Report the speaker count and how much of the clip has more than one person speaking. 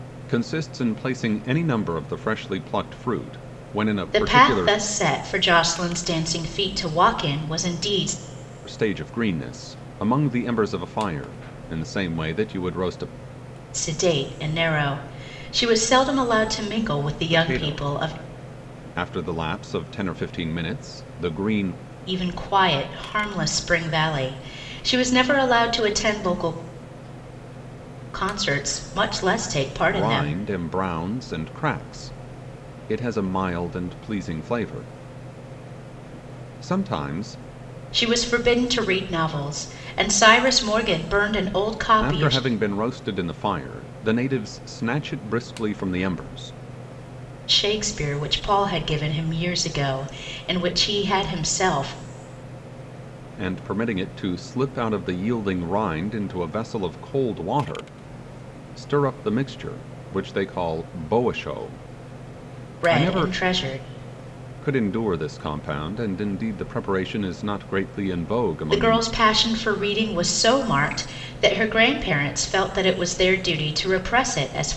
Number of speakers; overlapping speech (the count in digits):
2, about 5%